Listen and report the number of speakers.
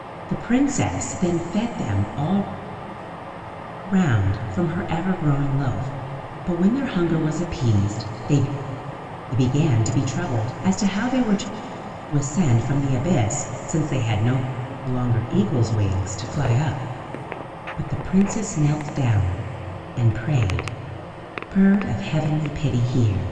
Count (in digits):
1